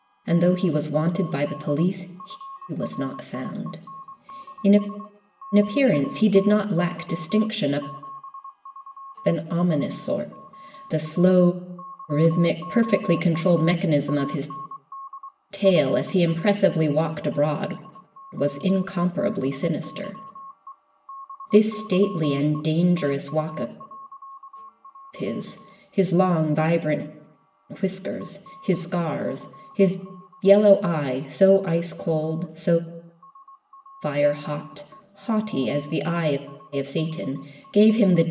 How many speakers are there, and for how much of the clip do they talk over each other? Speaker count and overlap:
1, no overlap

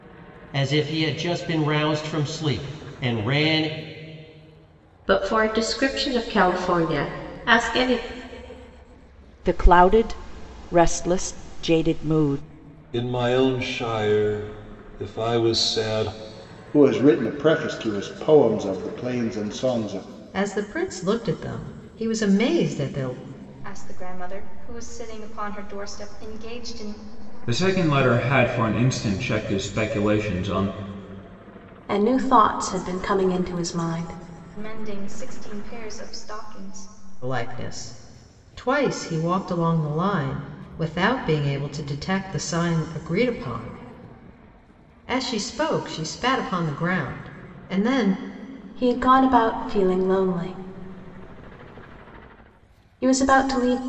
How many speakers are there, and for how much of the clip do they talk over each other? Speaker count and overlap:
9, no overlap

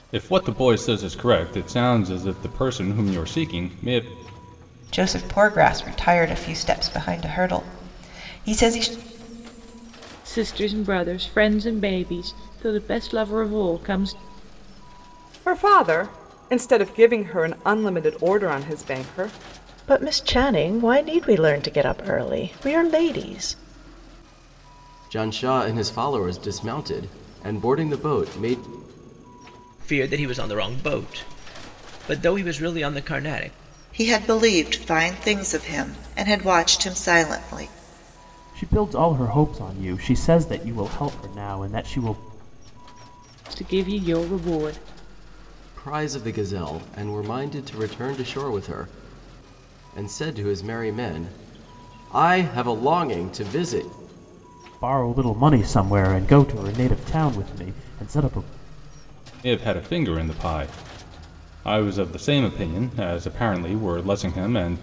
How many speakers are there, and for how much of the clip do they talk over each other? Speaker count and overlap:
9, no overlap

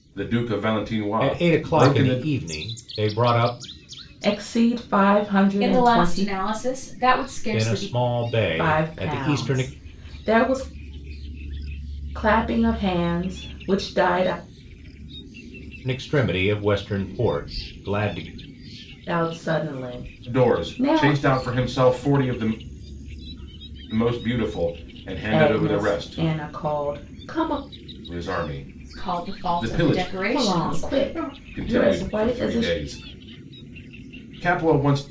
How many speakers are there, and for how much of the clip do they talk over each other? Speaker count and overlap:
4, about 25%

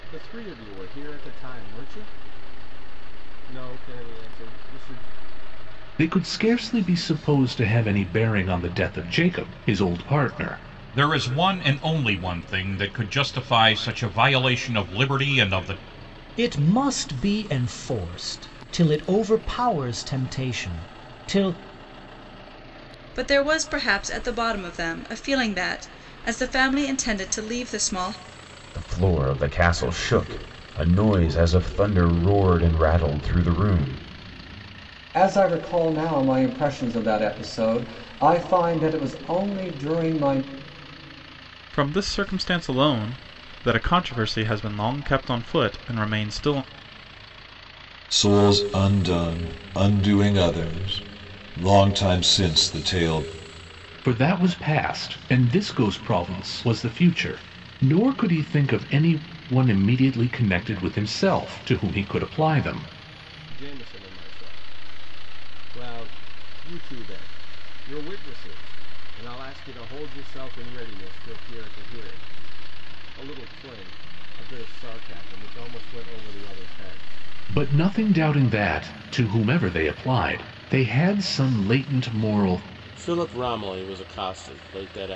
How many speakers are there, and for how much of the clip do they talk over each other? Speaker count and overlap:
9, no overlap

